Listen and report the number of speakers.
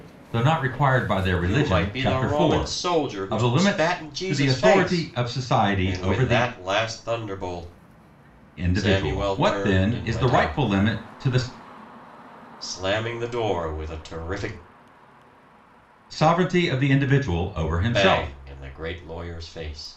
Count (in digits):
2